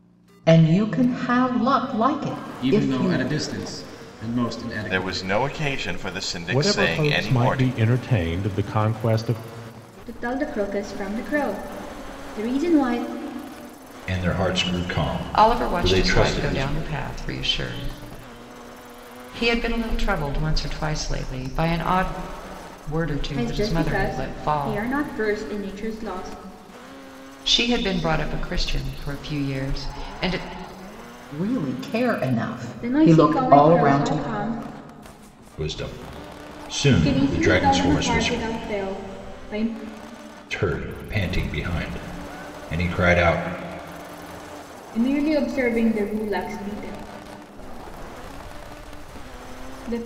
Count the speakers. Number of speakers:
7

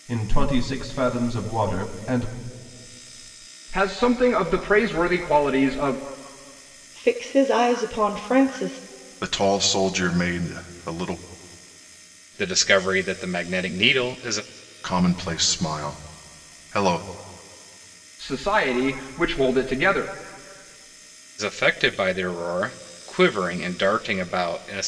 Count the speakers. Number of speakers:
5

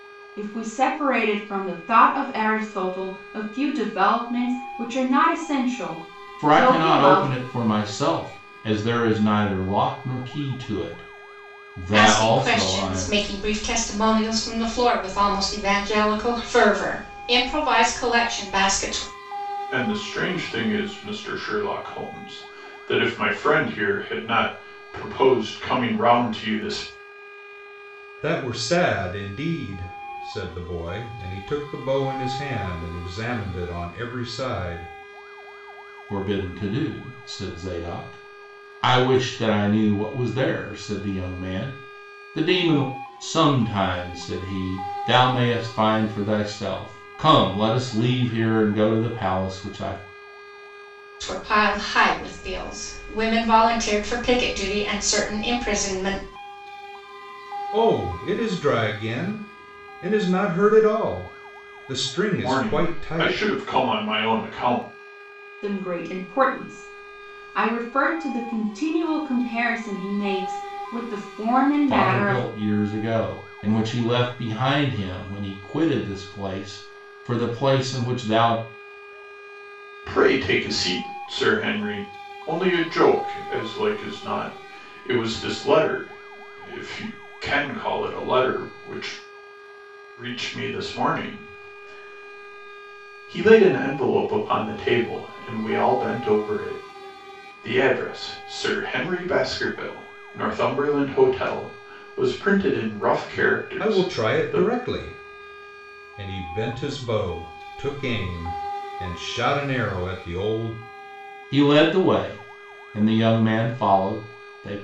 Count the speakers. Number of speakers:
5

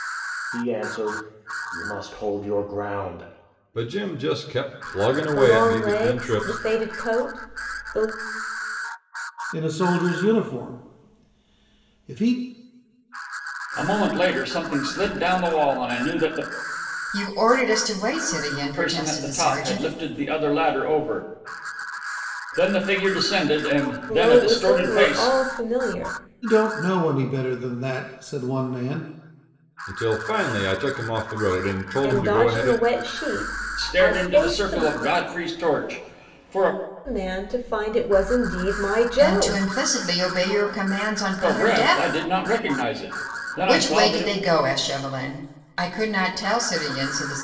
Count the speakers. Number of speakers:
6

